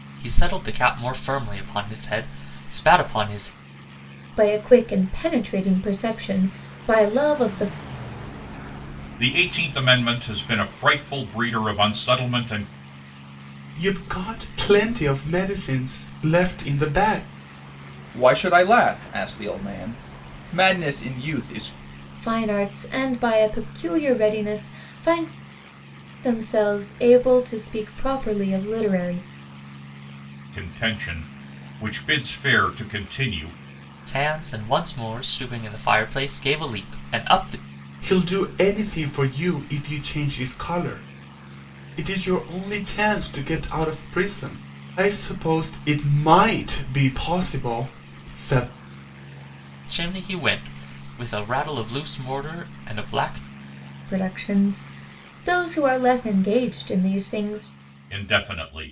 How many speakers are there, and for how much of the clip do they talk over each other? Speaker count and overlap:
5, no overlap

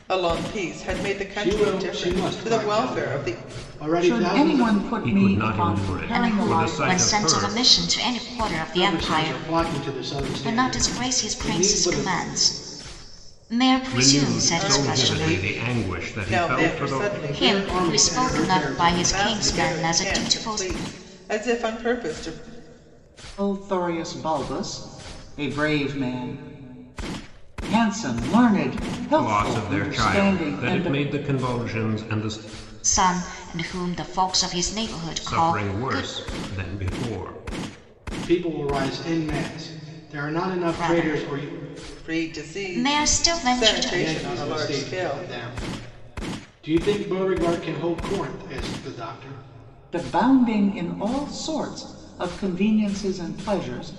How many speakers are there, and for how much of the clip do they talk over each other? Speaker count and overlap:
5, about 40%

